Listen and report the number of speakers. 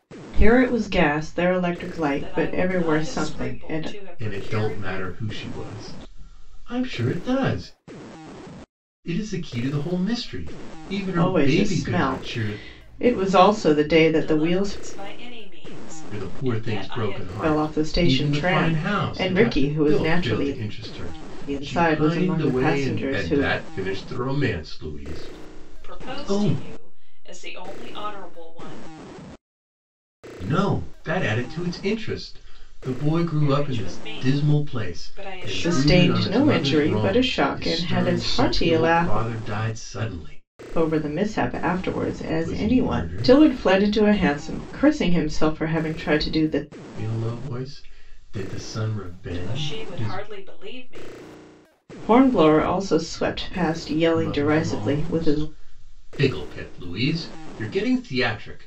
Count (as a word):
three